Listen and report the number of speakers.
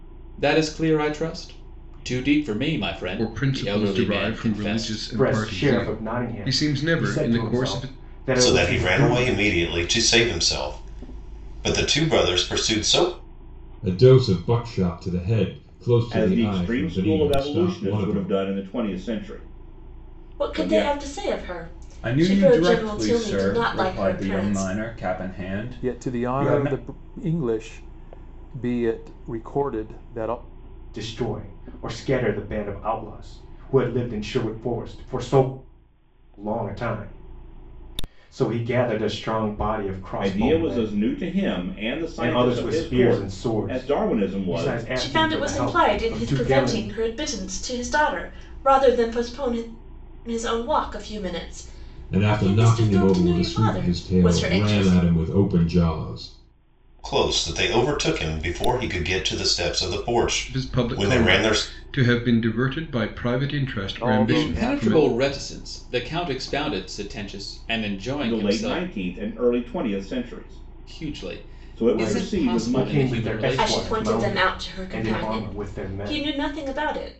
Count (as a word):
nine